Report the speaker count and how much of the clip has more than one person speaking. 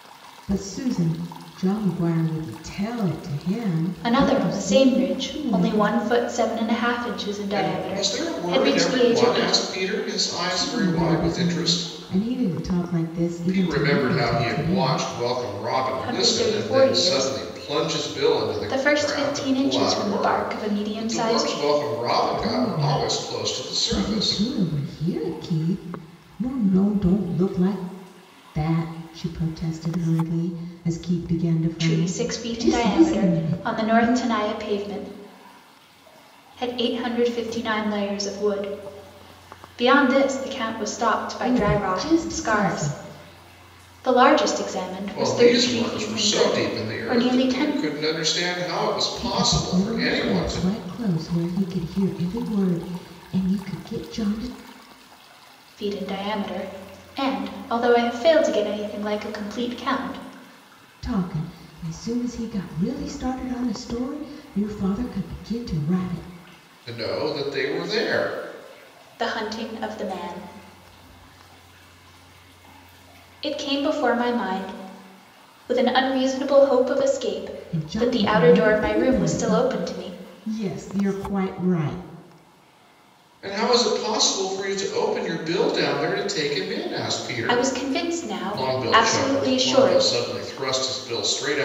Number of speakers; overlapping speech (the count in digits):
3, about 31%